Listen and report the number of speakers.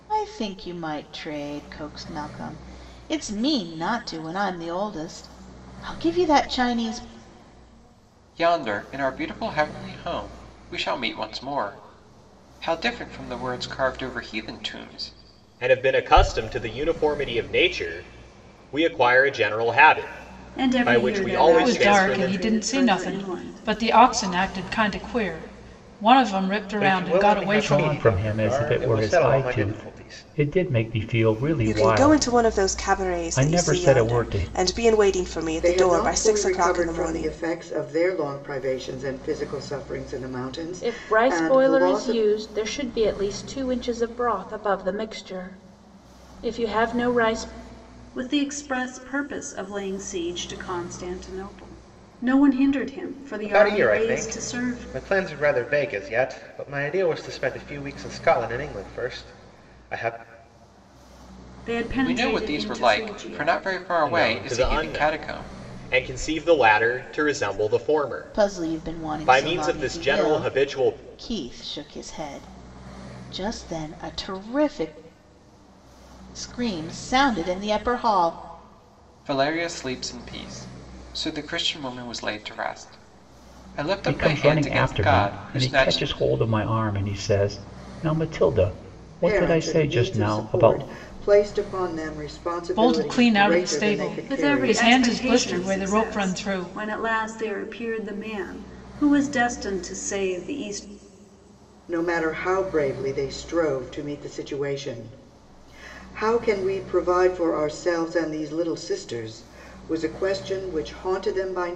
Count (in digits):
10